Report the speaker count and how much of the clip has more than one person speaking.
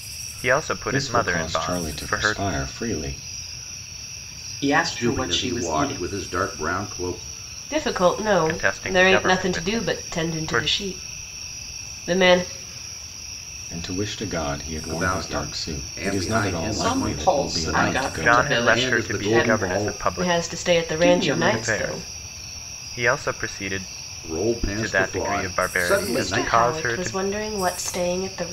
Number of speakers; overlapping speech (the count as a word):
five, about 52%